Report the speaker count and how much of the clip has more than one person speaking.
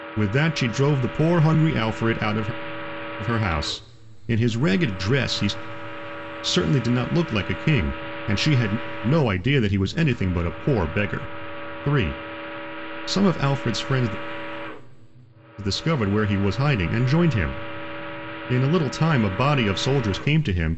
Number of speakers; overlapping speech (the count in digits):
1, no overlap